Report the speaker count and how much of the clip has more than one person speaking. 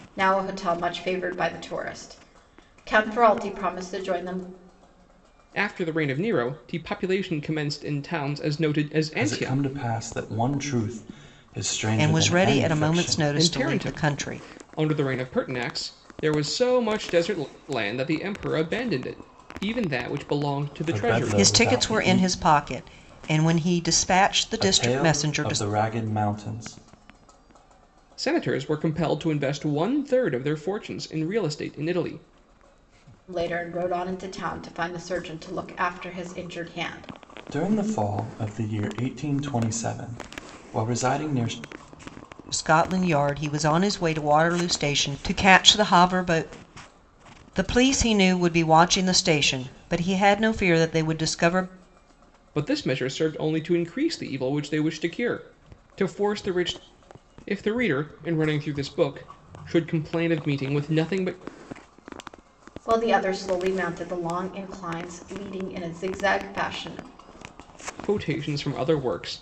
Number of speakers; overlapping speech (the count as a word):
four, about 8%